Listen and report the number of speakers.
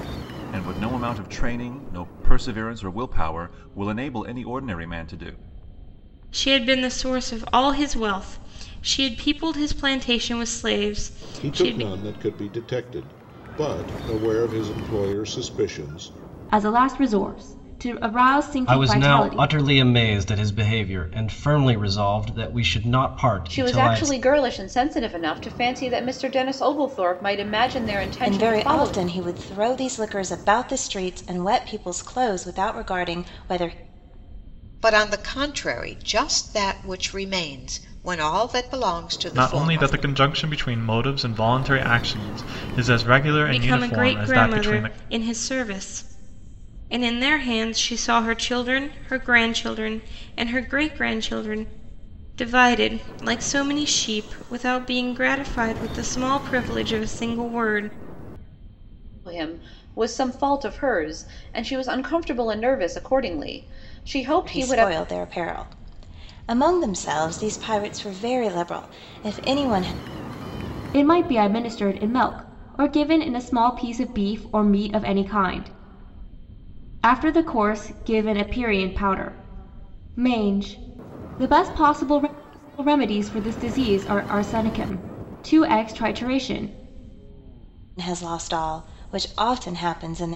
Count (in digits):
9